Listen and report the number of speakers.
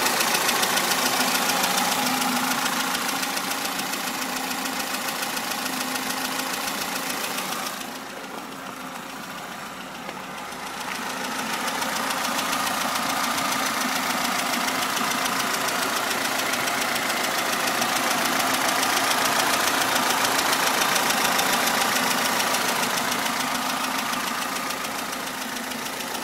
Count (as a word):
zero